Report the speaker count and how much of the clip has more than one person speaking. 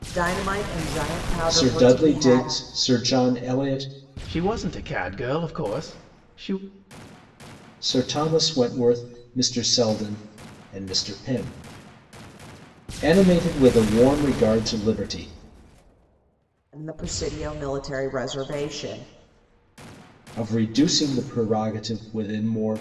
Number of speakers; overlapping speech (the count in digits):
3, about 5%